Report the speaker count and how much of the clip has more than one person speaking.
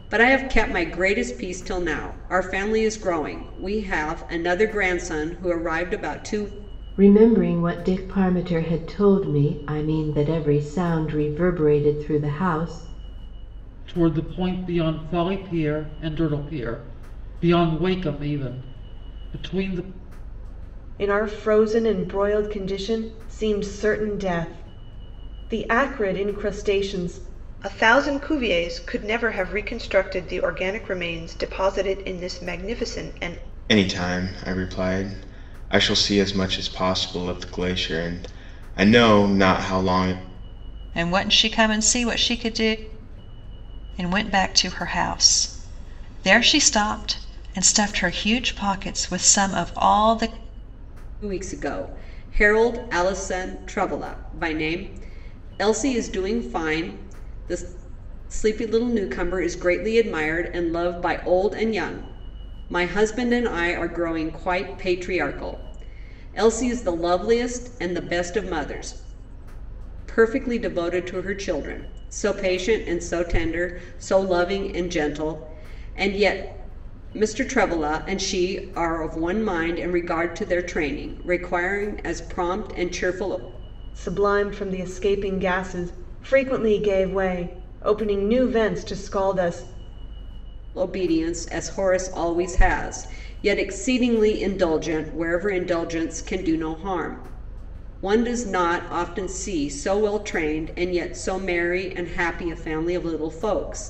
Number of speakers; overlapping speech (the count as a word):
seven, no overlap